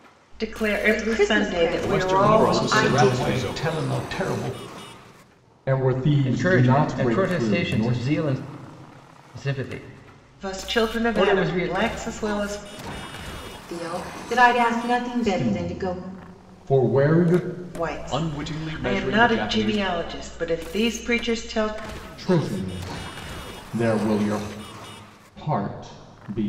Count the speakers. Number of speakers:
six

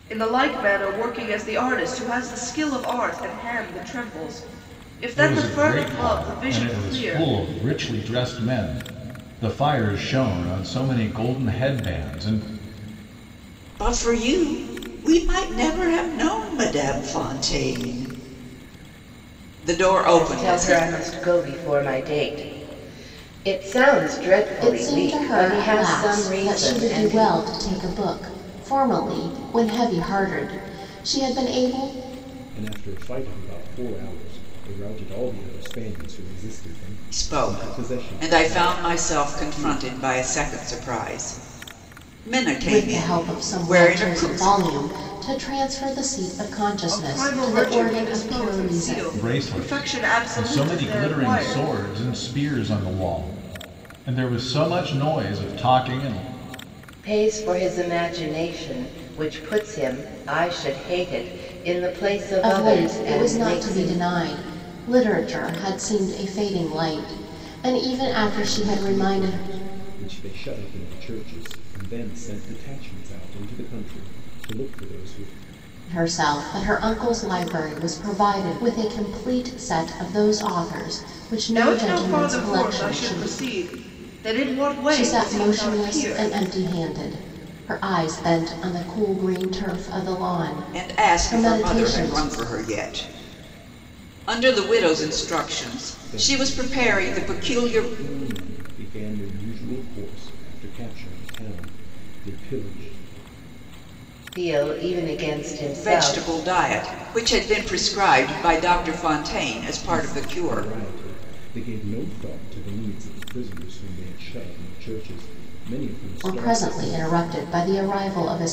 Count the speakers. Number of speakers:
six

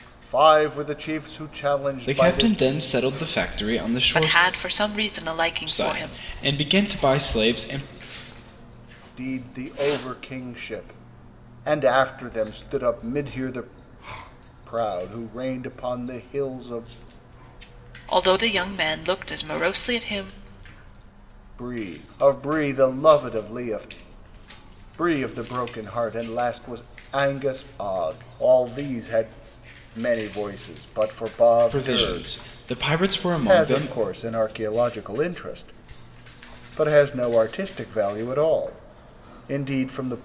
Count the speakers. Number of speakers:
three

